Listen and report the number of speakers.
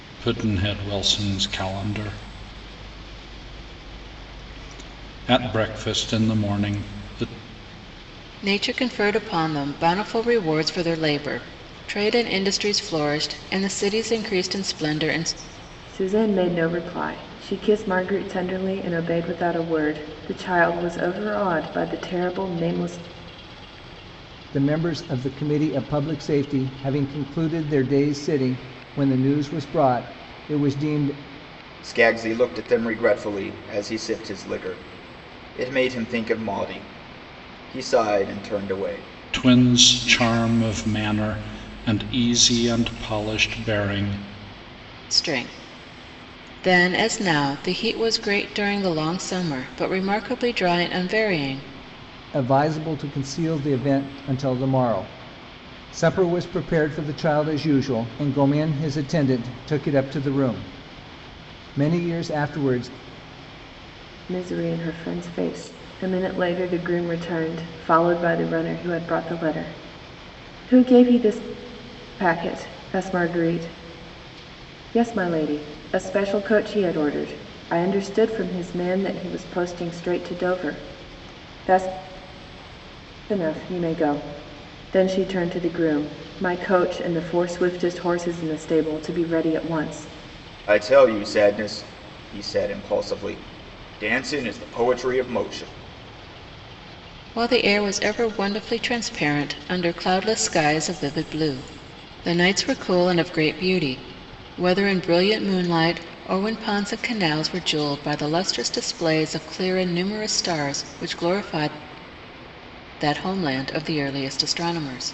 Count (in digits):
5